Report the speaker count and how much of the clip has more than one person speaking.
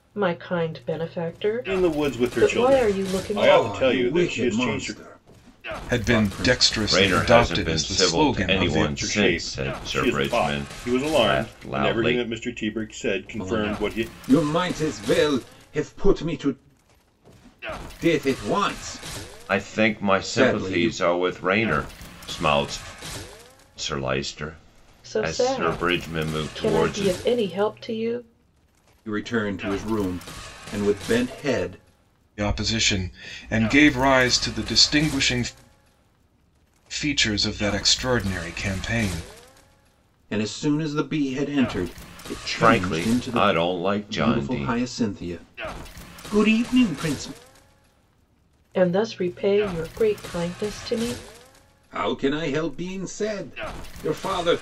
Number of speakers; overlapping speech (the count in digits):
5, about 28%